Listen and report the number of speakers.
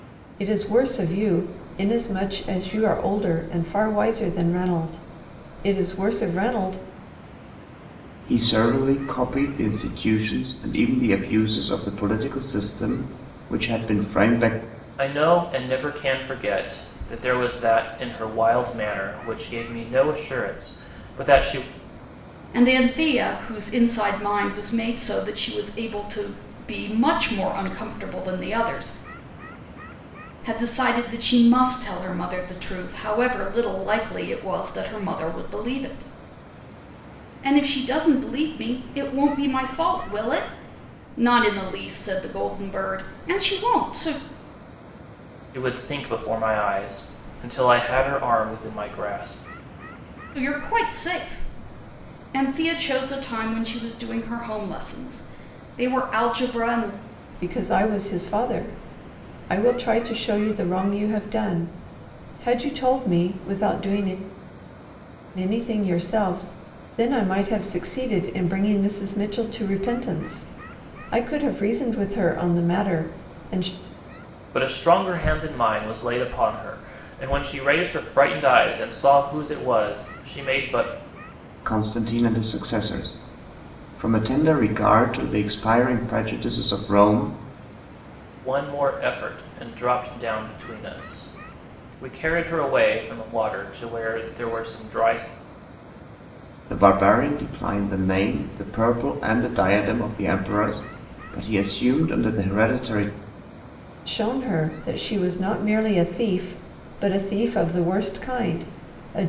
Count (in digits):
4